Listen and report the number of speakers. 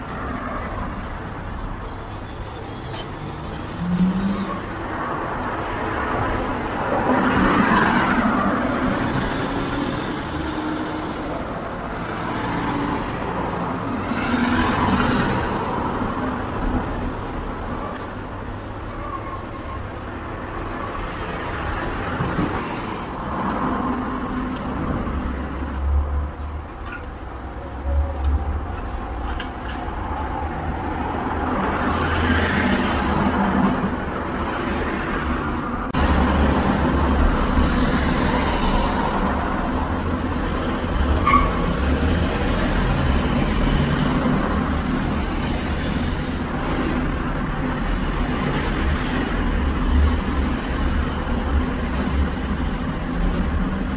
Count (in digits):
0